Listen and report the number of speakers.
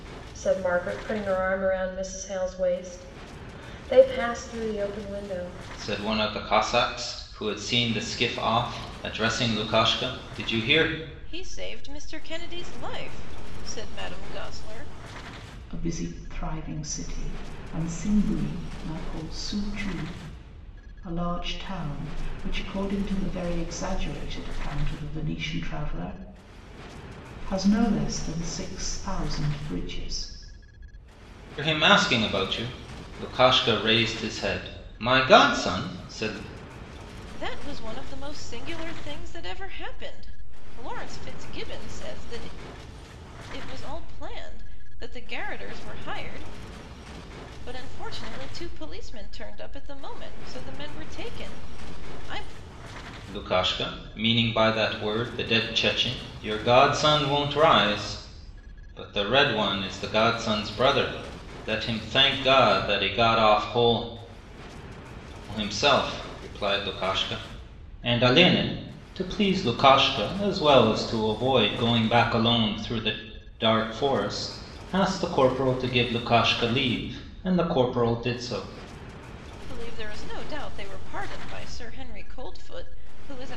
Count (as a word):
four